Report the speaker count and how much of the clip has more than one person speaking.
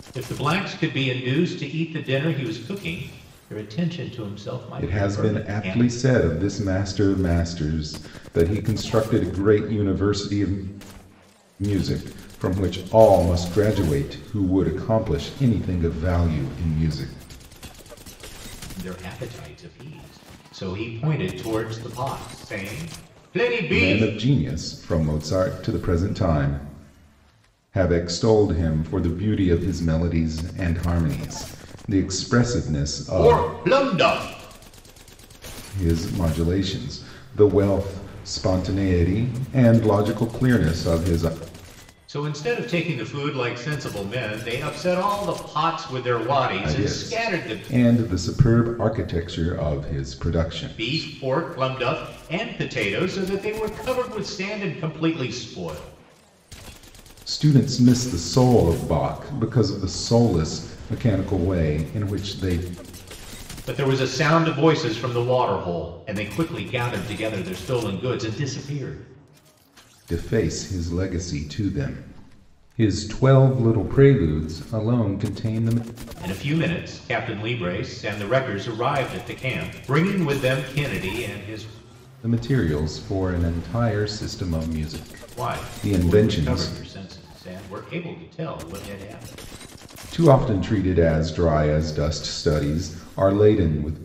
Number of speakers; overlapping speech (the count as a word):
two, about 5%